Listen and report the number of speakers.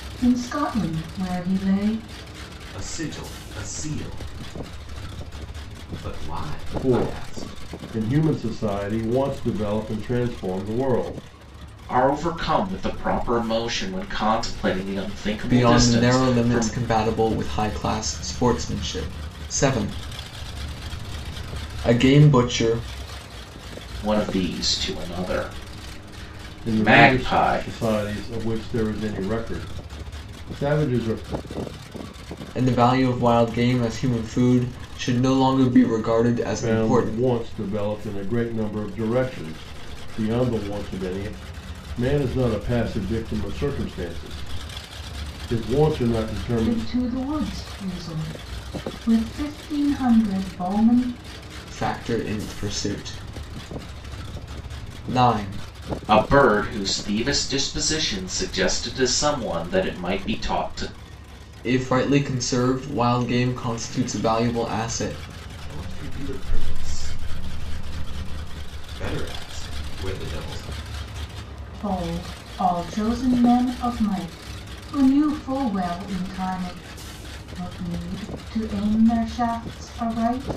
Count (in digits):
5